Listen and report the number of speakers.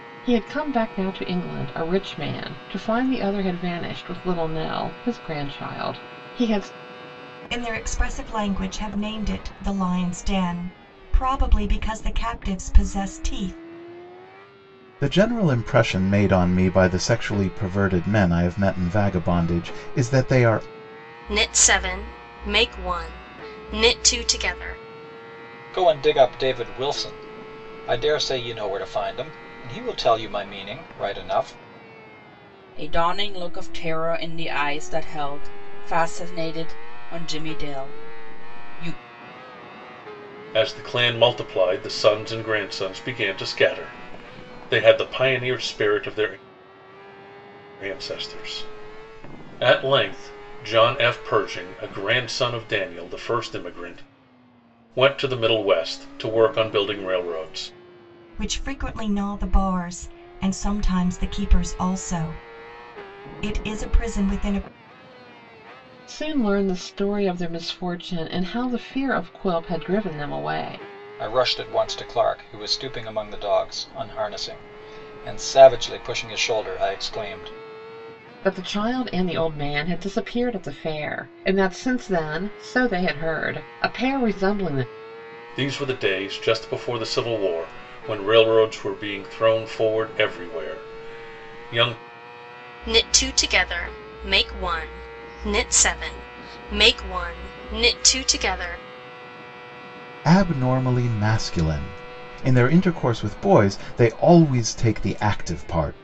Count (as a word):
seven